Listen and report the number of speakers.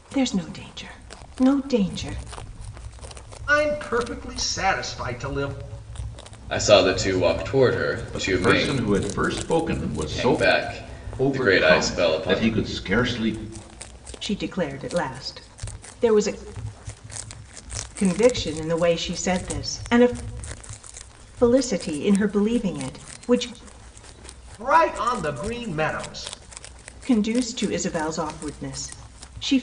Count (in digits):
4